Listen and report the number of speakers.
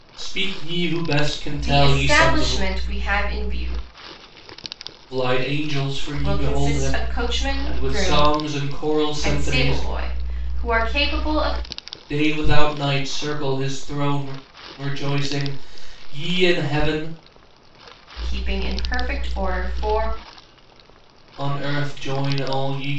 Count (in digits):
2